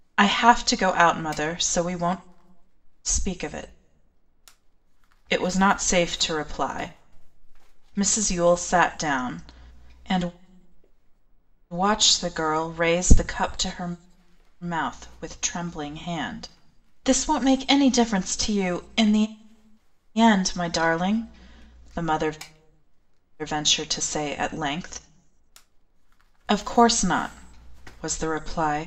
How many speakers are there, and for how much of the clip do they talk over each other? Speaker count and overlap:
1, no overlap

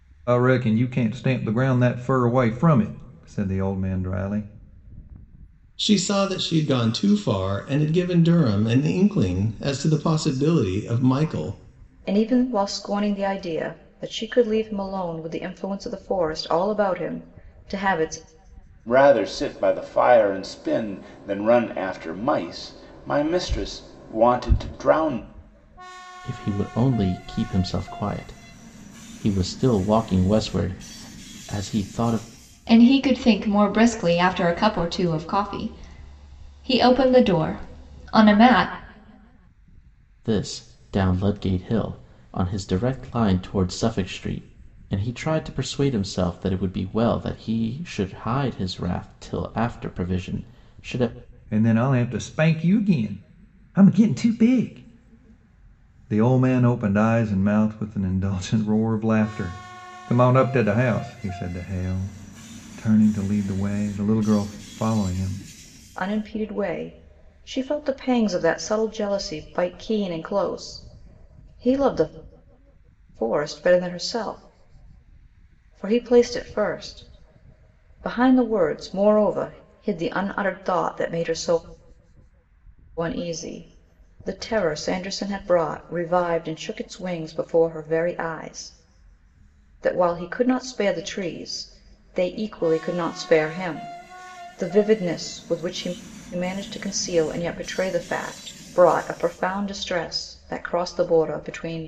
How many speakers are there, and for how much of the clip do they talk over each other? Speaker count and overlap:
6, no overlap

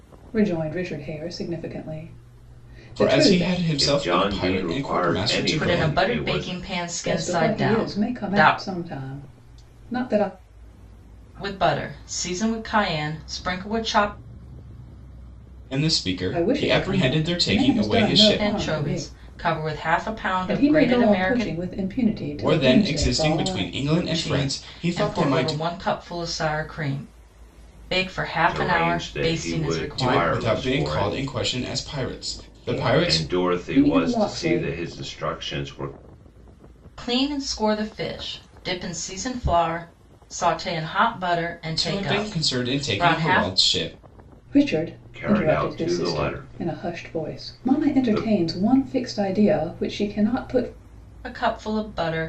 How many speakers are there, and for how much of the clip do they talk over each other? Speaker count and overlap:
4, about 41%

